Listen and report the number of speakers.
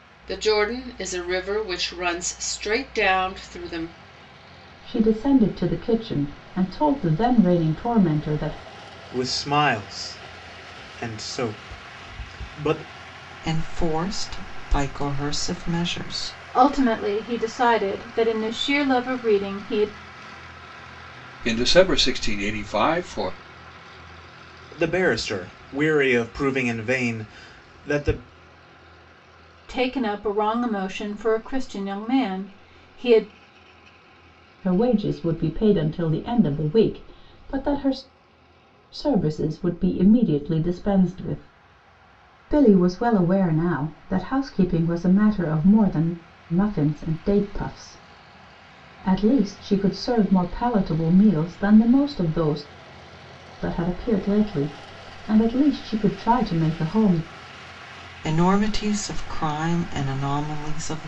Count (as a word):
six